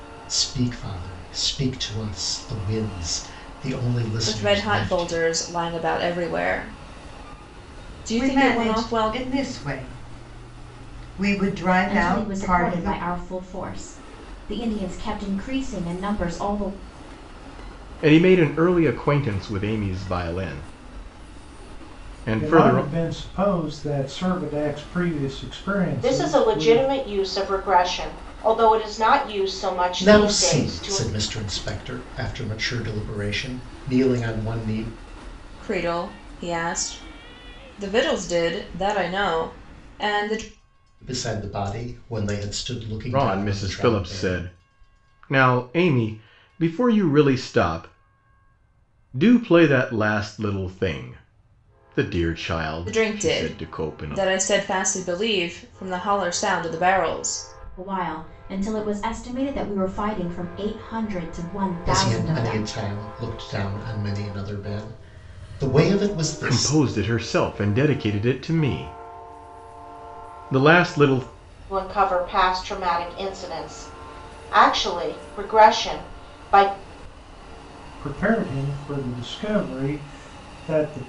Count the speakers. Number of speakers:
7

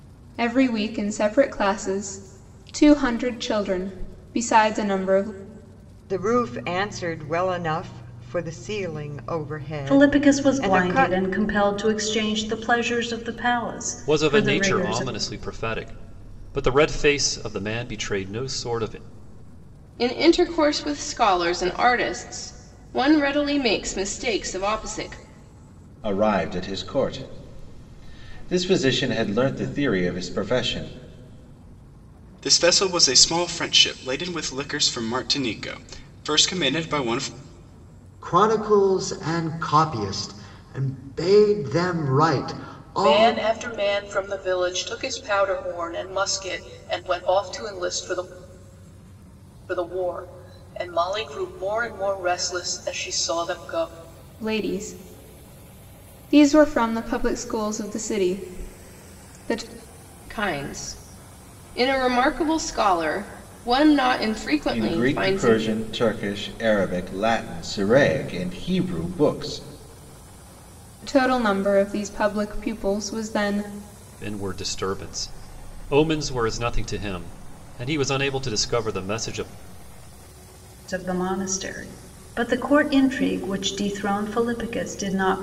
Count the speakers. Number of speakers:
9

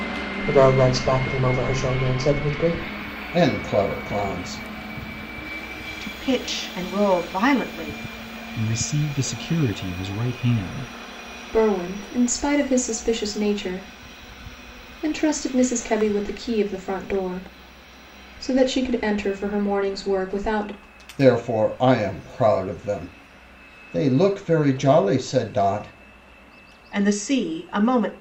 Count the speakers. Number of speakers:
5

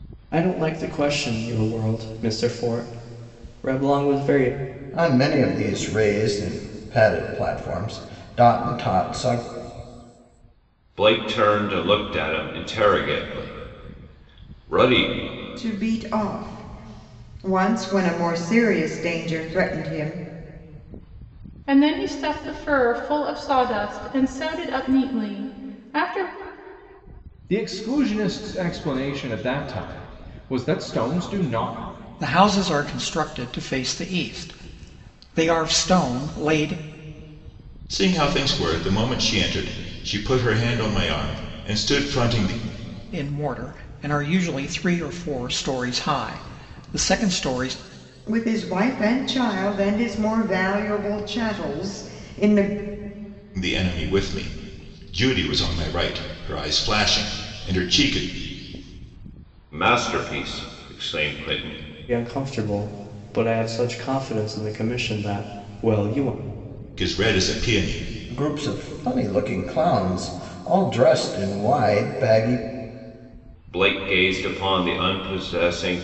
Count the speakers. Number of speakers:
8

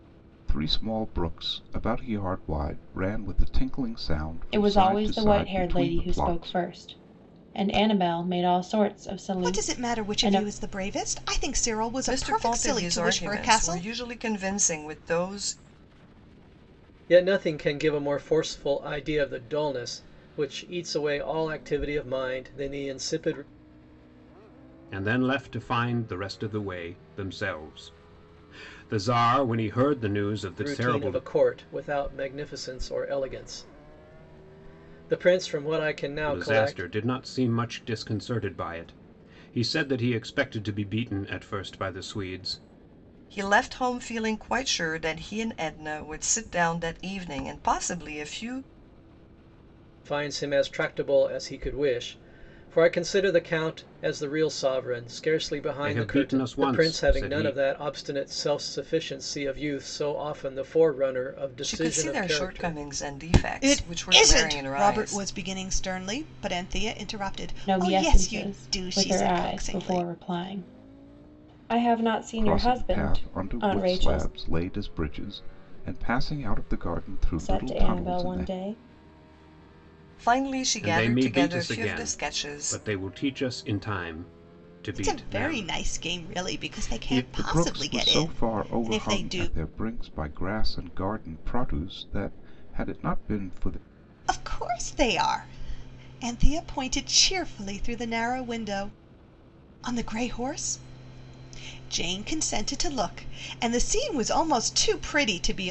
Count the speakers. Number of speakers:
6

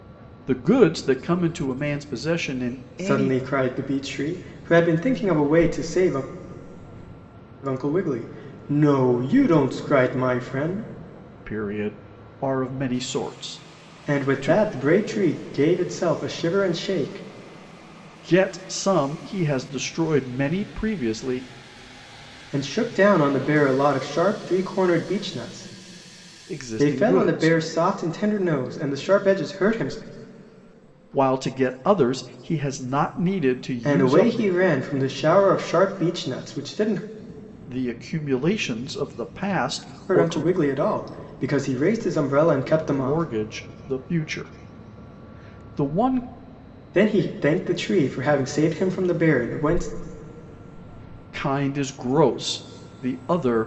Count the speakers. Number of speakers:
2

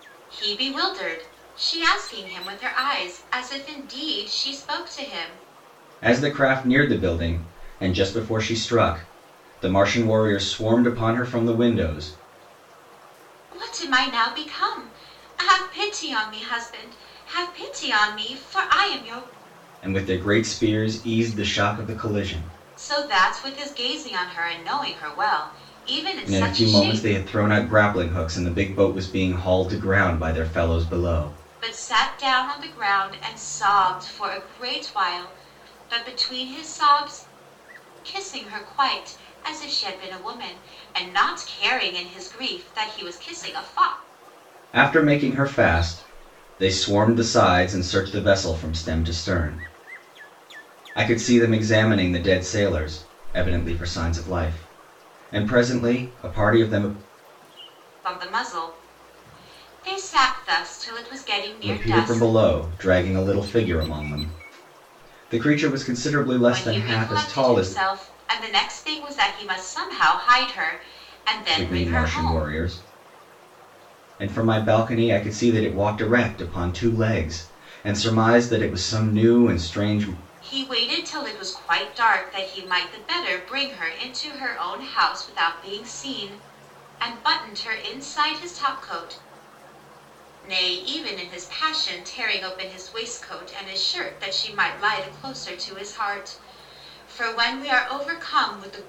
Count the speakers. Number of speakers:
2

